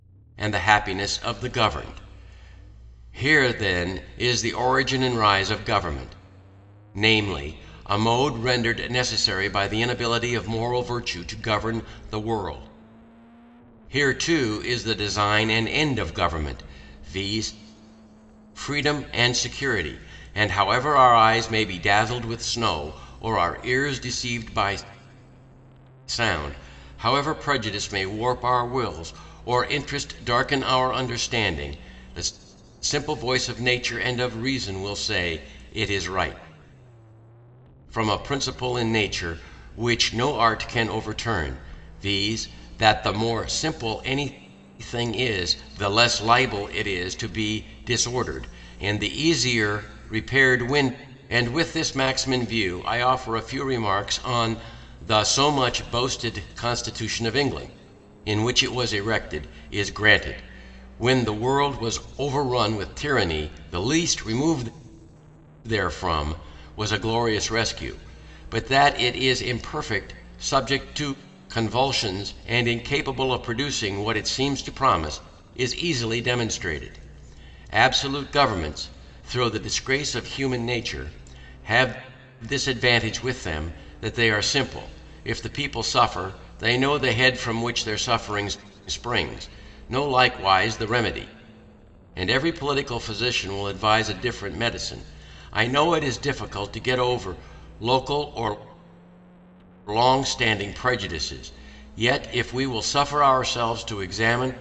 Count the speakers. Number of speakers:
one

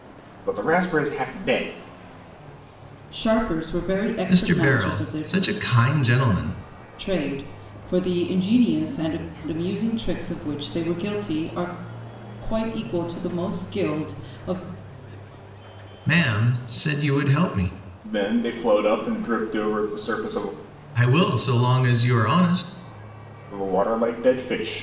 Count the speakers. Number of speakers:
three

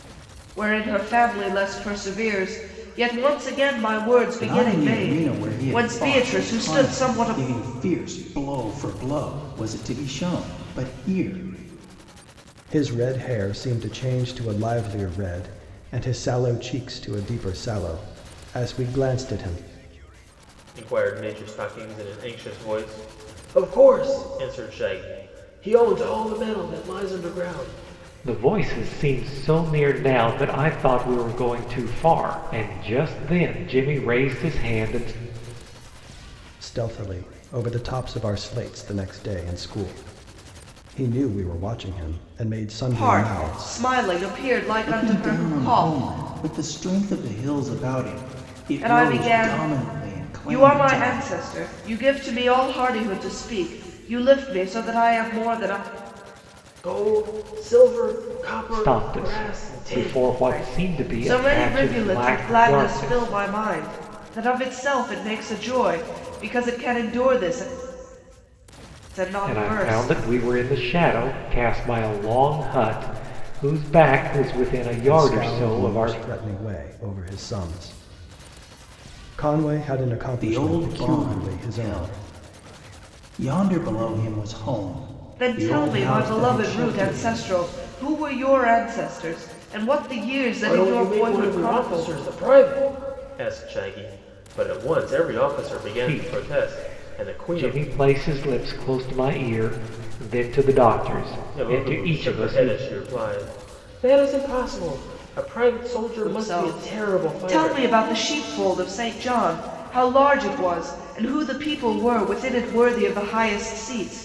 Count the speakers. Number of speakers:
five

